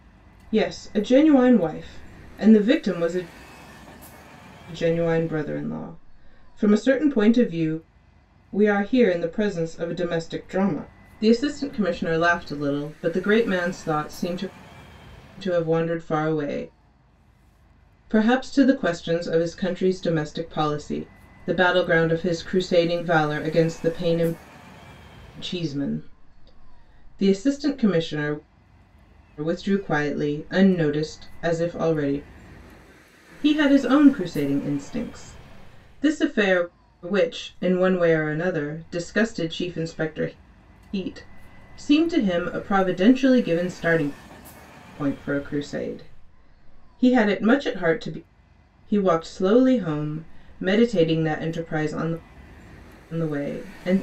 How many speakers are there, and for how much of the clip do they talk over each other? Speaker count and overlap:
one, no overlap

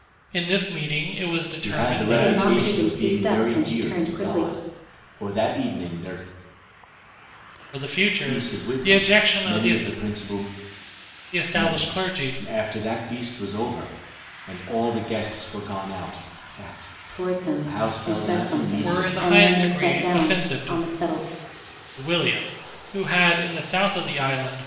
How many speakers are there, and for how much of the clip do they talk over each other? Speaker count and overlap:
three, about 35%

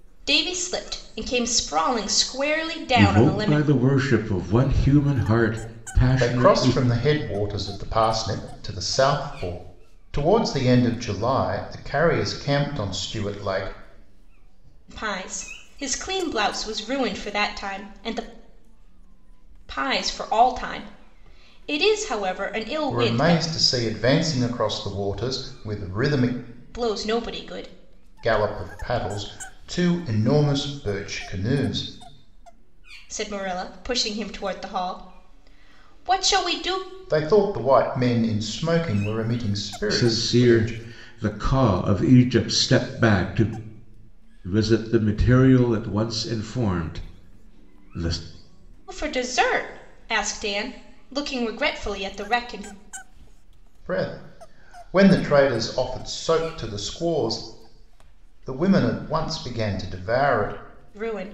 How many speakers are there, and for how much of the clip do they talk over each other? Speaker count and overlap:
three, about 5%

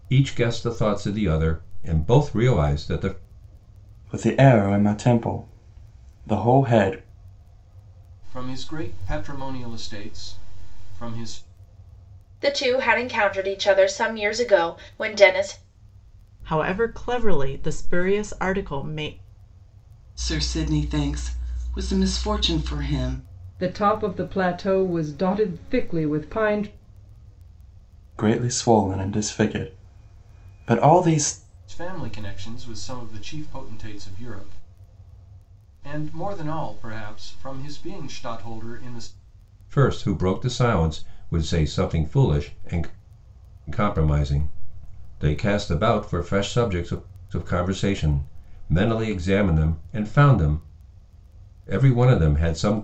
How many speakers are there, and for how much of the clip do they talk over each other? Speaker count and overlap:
seven, no overlap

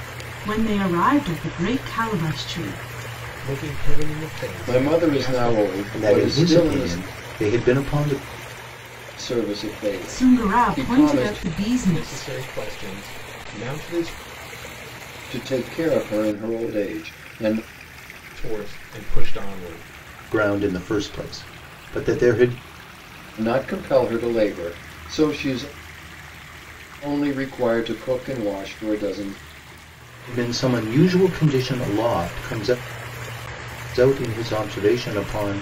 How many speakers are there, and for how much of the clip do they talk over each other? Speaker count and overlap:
four, about 11%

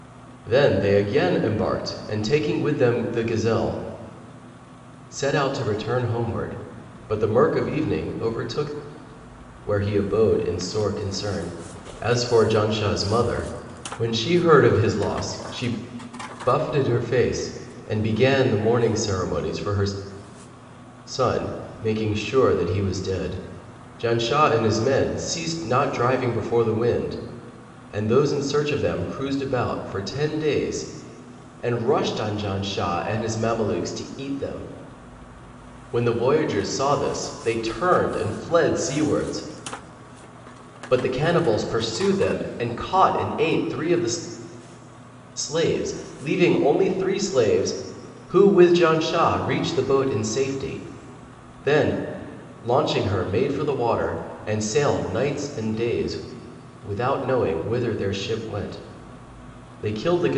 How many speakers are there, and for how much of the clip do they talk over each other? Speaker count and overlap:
one, no overlap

